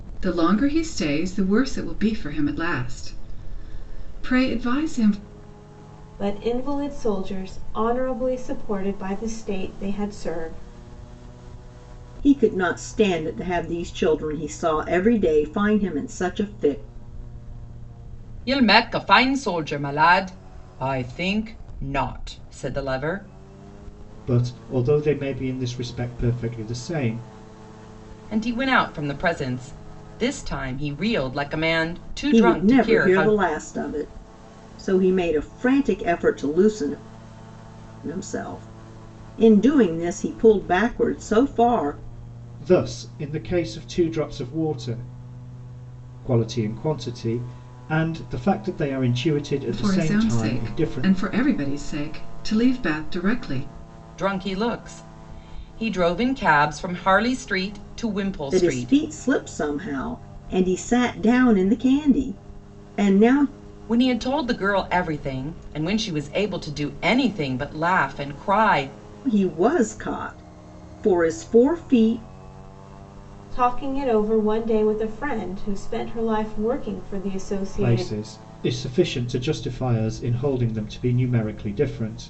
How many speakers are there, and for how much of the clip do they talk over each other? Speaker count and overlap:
5, about 4%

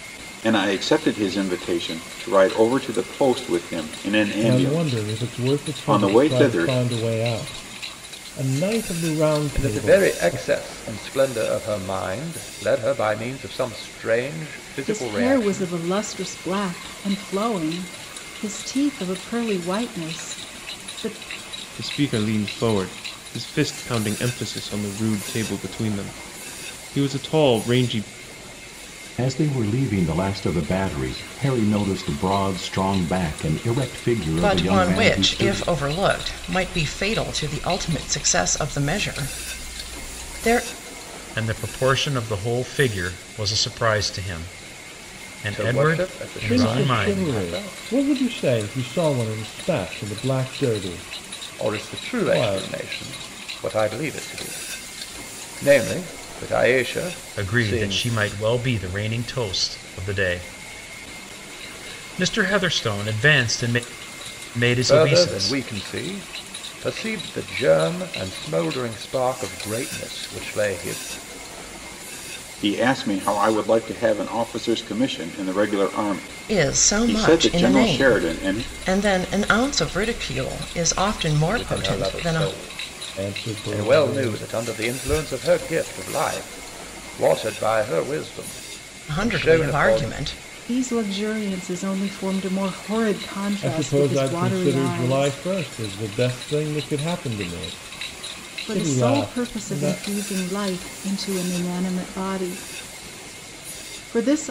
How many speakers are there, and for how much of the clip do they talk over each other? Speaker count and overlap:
8, about 18%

